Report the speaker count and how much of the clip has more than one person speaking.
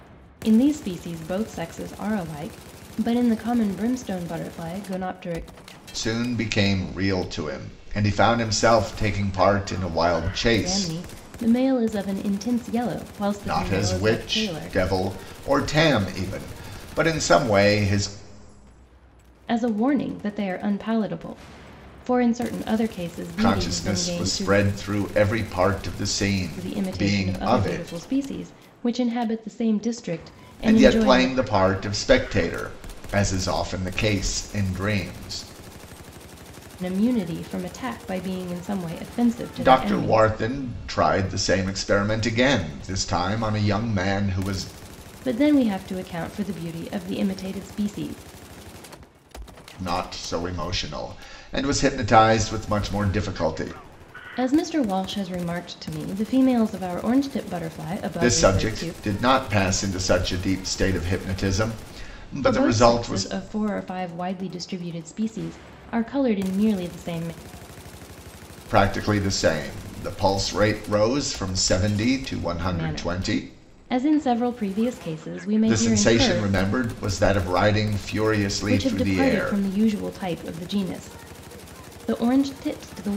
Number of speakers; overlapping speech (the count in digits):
2, about 12%